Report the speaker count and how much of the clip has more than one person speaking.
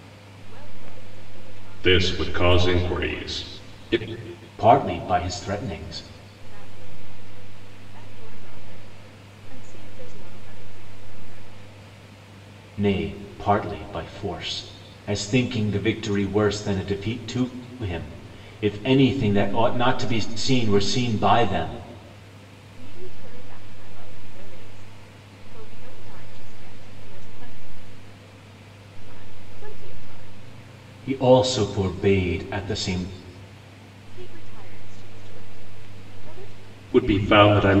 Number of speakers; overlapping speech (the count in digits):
3, about 8%